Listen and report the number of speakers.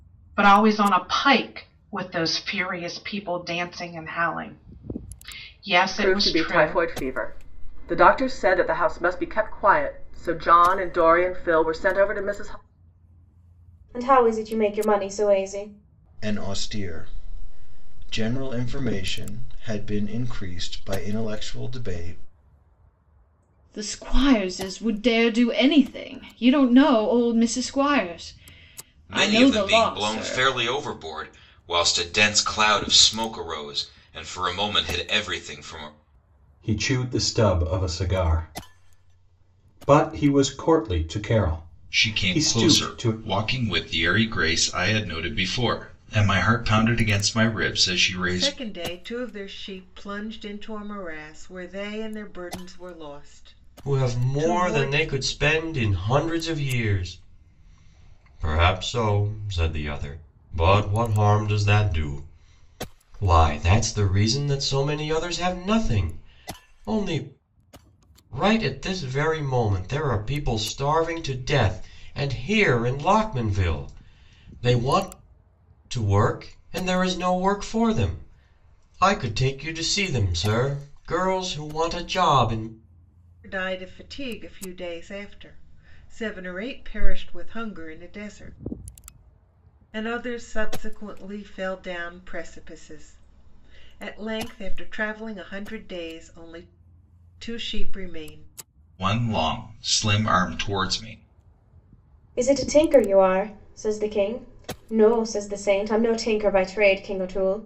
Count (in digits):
10